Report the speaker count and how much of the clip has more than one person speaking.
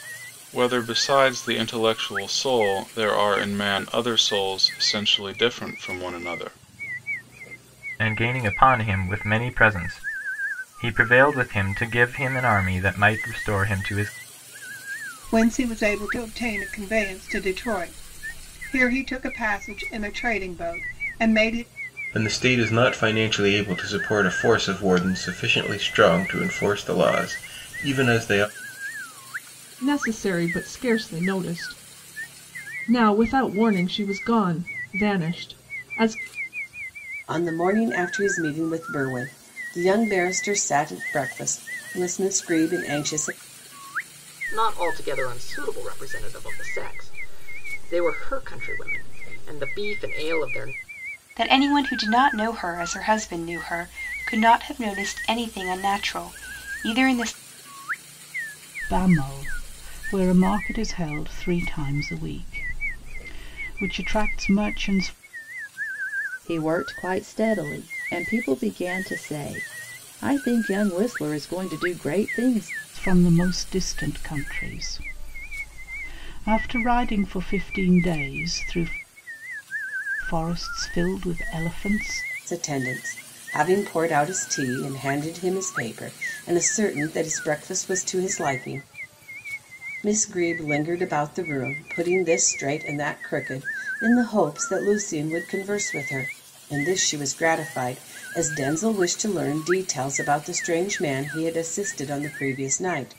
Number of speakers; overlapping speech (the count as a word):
ten, no overlap